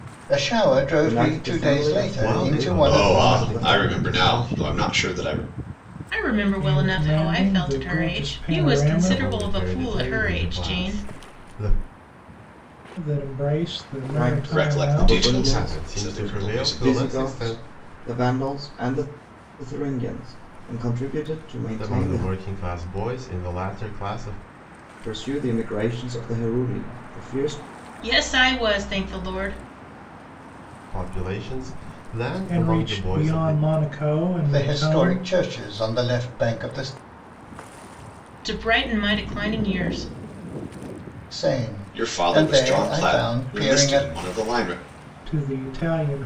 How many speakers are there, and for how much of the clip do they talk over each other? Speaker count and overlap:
6, about 36%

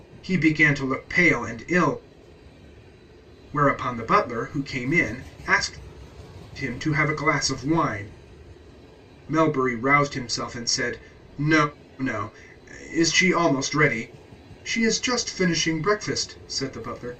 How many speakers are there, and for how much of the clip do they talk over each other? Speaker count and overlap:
1, no overlap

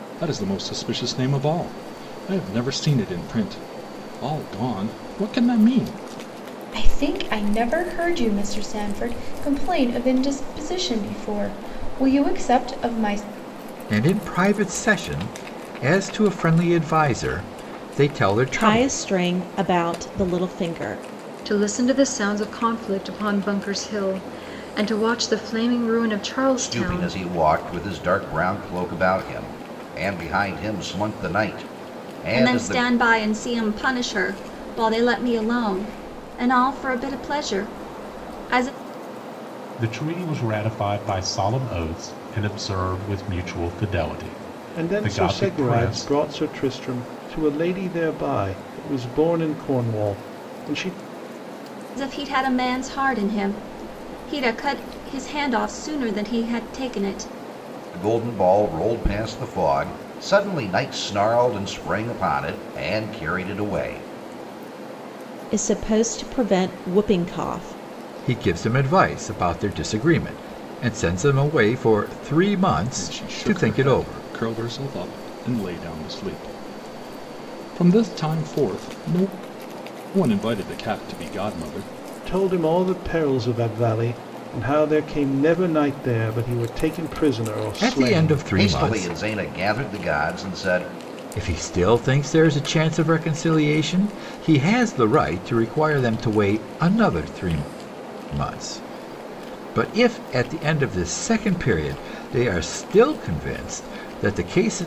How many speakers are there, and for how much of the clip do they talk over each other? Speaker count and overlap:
9, about 6%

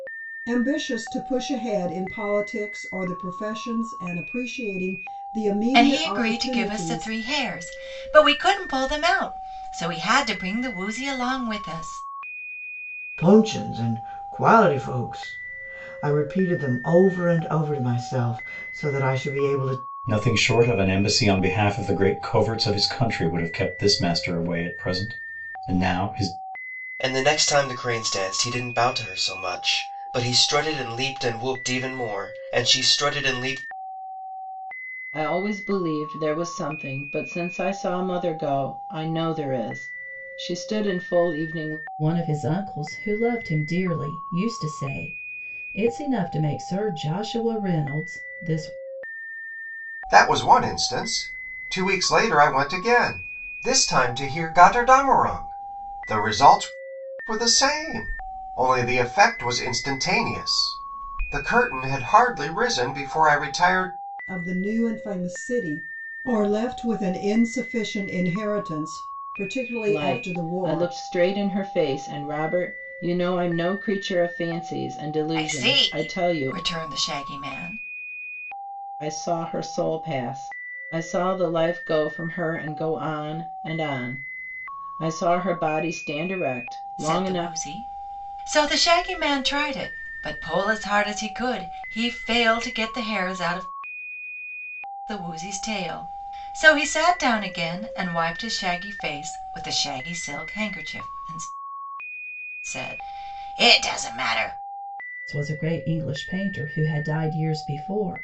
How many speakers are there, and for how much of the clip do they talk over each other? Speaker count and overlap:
8, about 4%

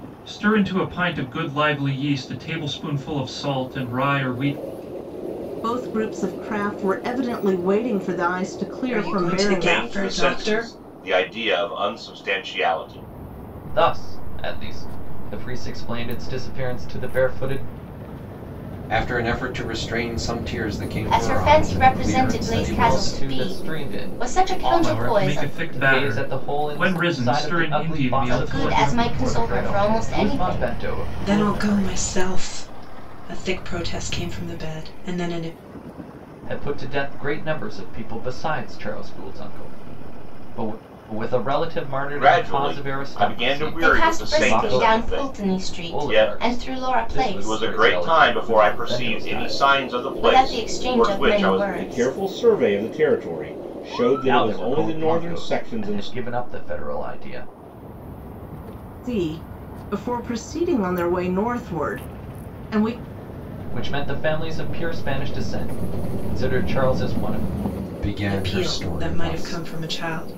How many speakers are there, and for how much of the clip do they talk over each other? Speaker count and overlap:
7, about 35%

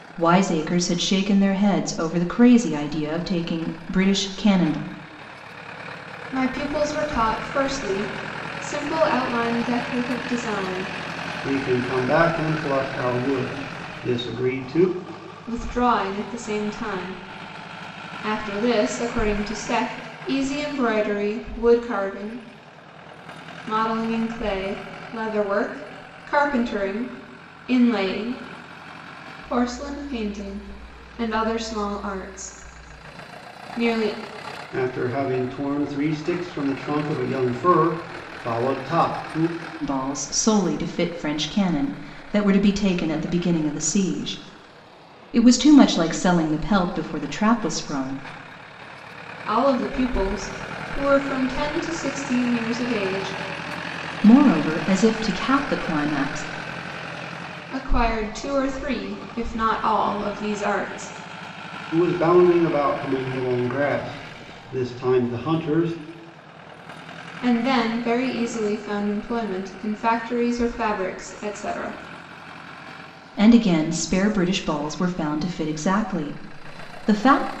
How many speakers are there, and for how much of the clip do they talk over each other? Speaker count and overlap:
3, no overlap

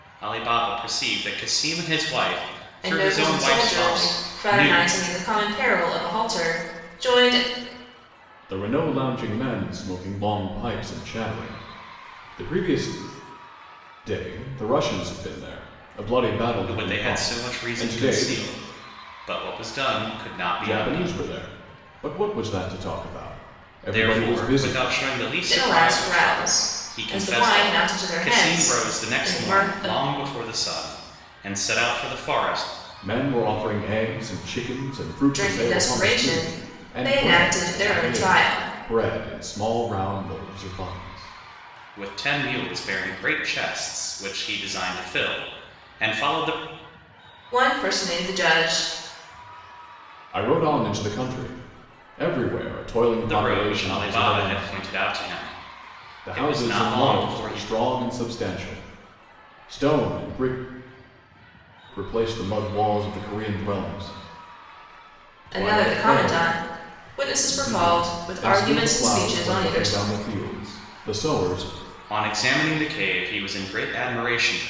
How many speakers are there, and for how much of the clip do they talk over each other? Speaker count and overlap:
3, about 26%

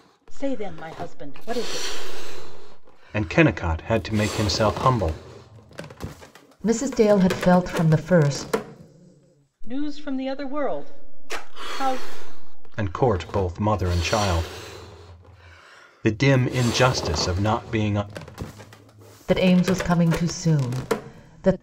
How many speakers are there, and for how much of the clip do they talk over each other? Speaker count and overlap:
3, no overlap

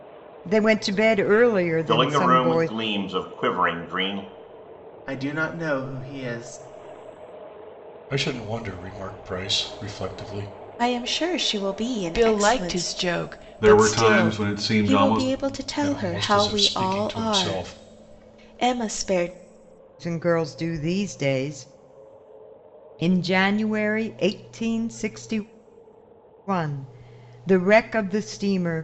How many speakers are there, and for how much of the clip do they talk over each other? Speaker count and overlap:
7, about 18%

